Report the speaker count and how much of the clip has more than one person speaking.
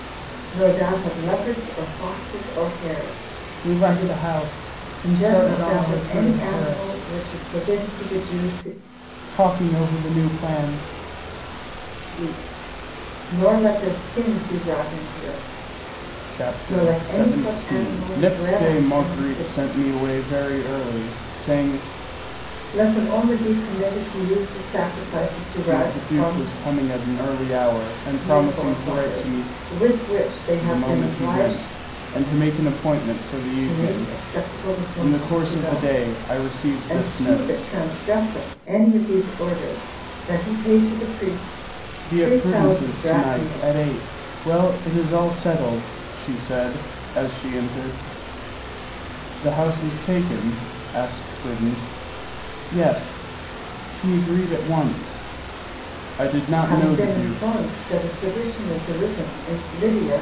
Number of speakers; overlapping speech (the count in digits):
2, about 24%